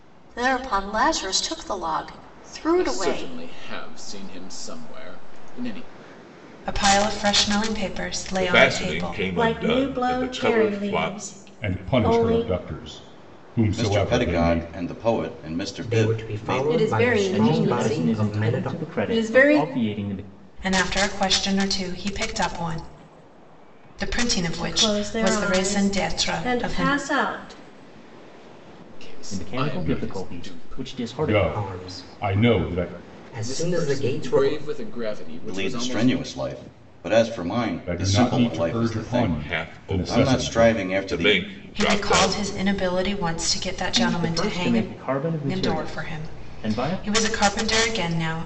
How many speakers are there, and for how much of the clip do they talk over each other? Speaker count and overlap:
ten, about 49%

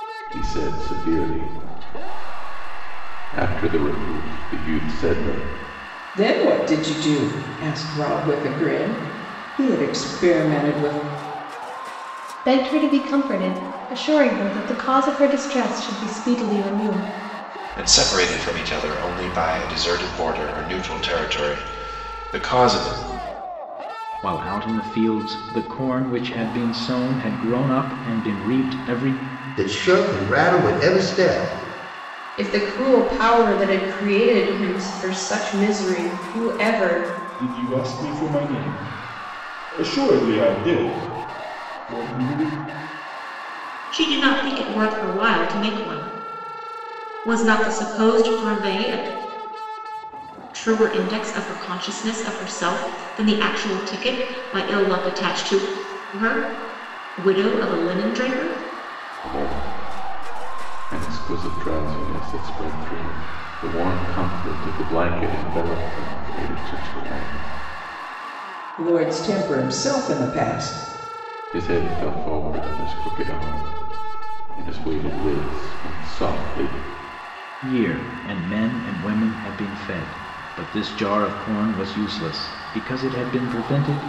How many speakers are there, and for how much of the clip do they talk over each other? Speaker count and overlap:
nine, no overlap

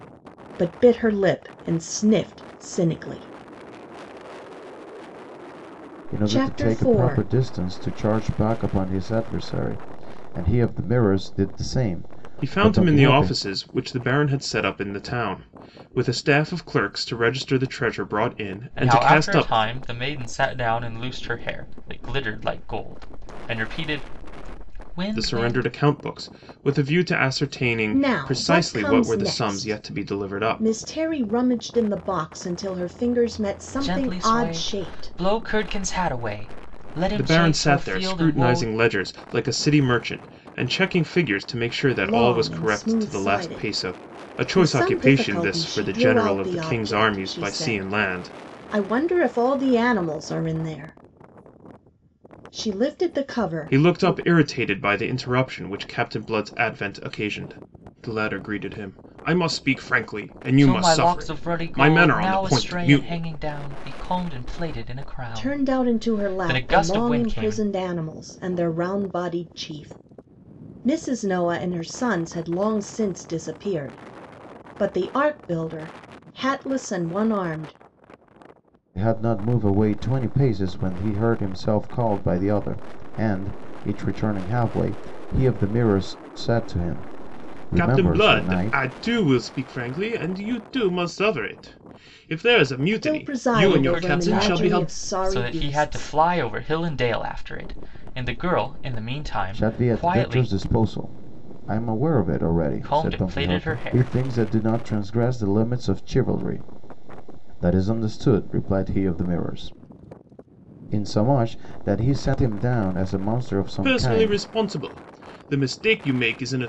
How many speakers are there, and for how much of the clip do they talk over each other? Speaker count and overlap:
four, about 24%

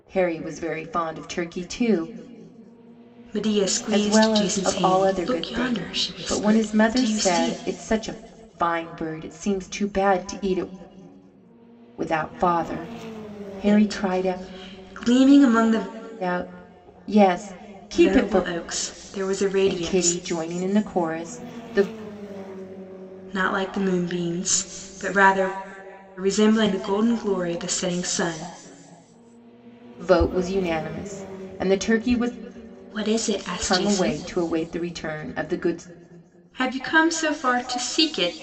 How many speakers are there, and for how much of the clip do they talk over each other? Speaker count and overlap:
two, about 16%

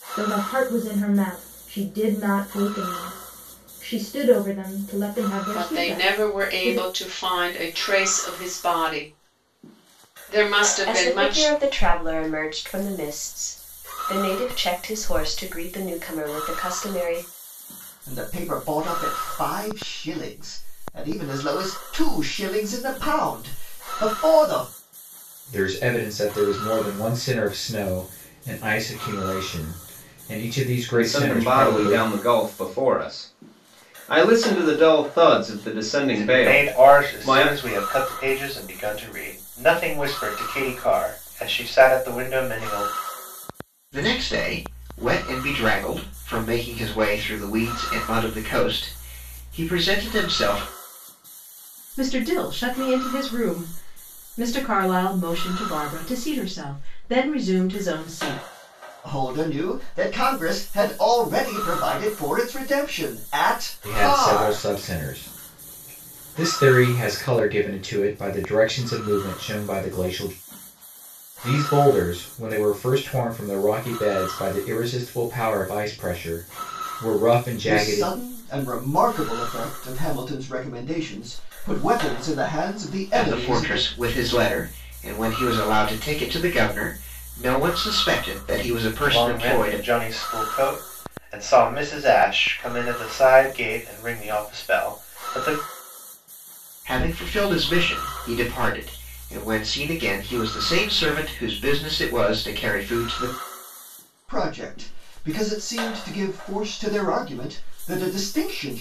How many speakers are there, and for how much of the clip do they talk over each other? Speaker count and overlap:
nine, about 7%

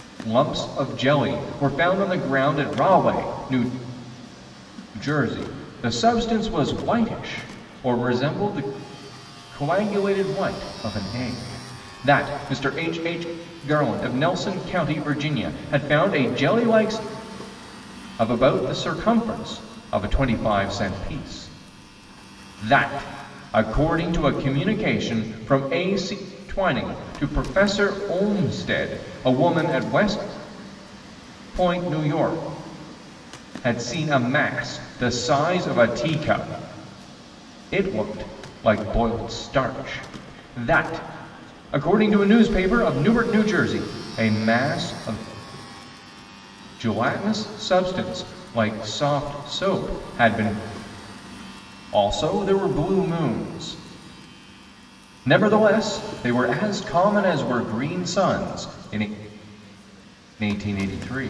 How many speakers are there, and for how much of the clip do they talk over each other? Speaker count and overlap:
one, no overlap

